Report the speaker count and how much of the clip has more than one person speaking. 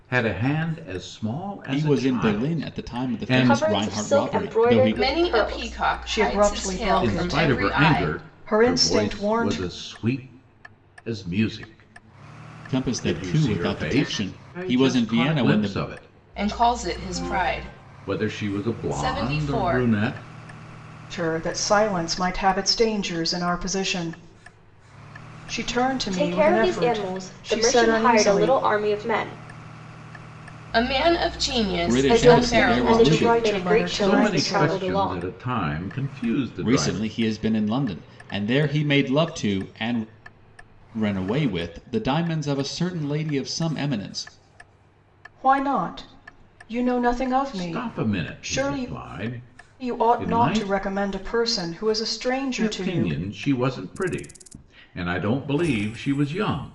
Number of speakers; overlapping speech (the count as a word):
five, about 39%